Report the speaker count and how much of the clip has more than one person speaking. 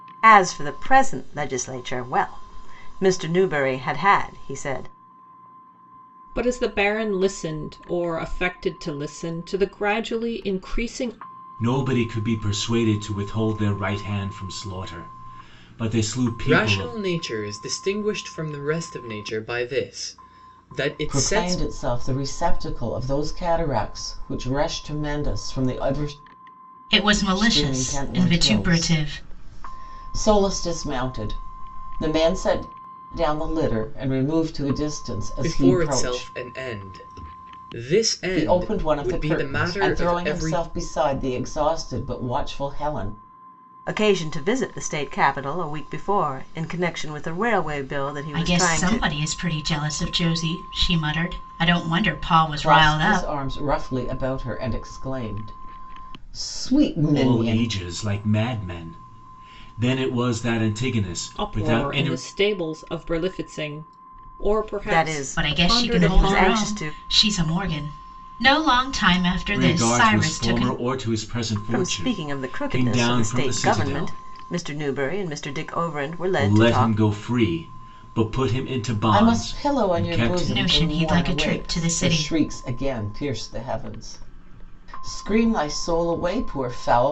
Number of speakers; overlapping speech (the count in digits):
6, about 22%